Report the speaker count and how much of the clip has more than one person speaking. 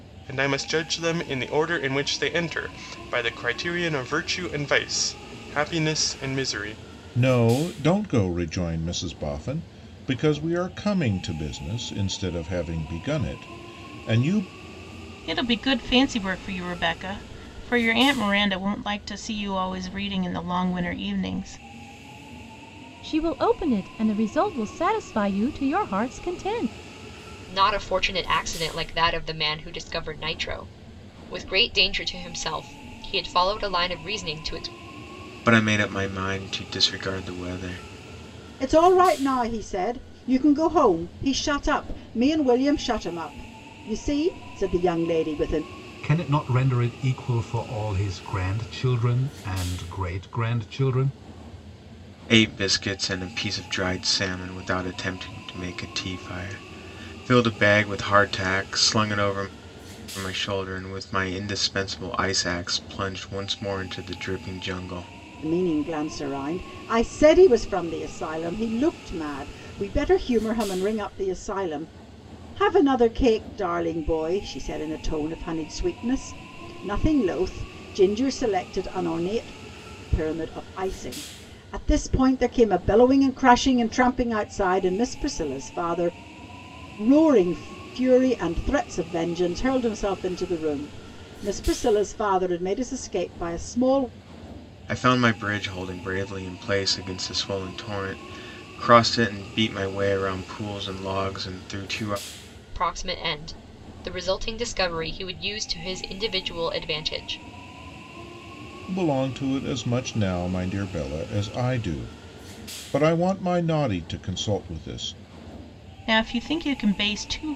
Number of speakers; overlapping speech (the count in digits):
8, no overlap